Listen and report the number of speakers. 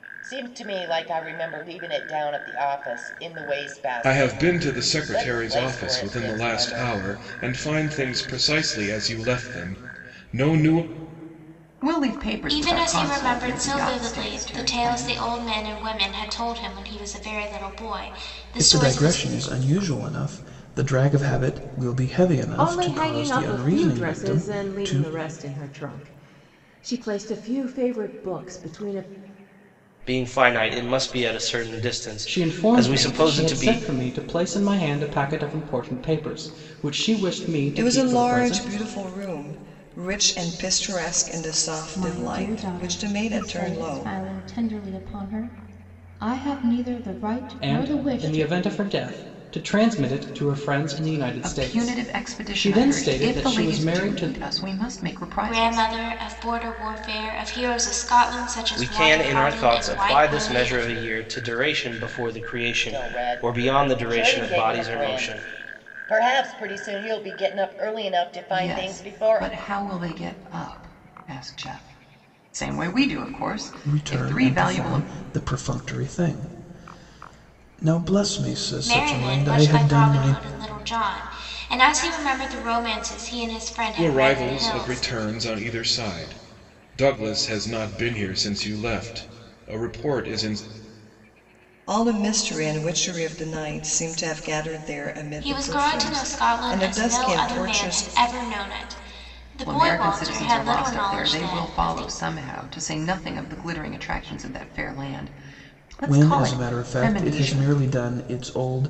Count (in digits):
10